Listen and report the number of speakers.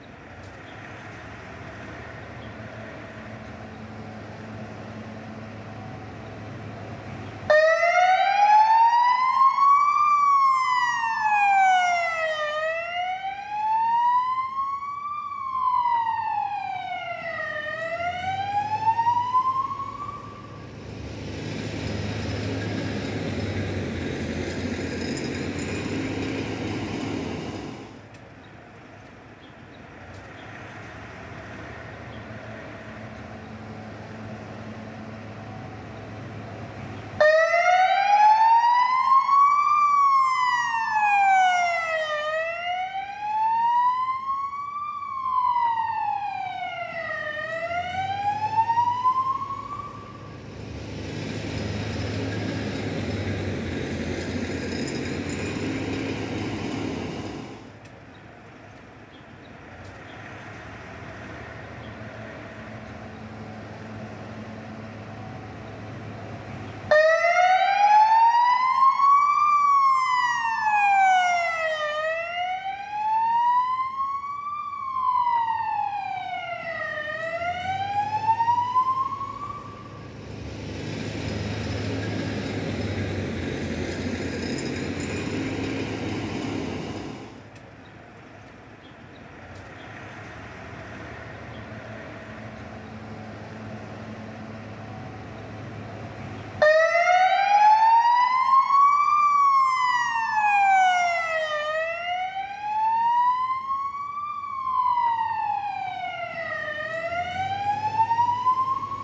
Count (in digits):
0